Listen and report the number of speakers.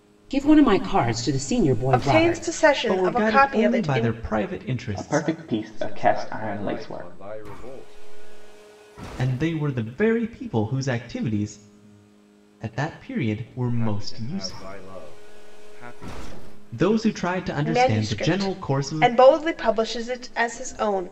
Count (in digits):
5